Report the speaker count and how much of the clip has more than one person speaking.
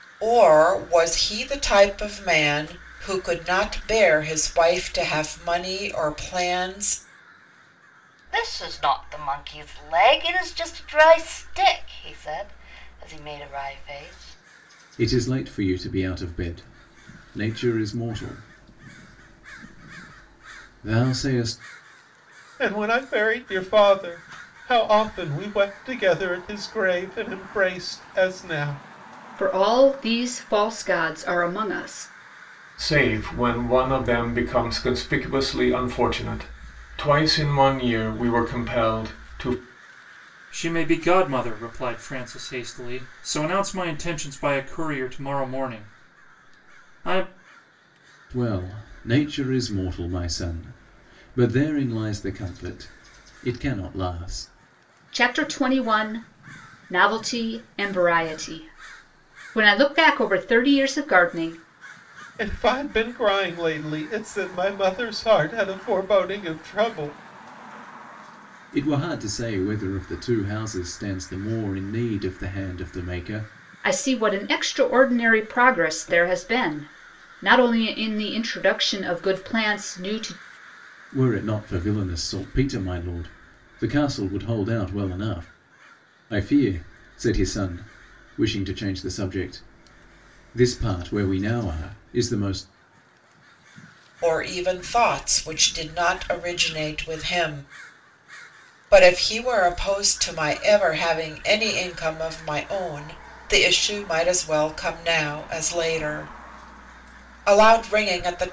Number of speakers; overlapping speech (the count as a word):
seven, no overlap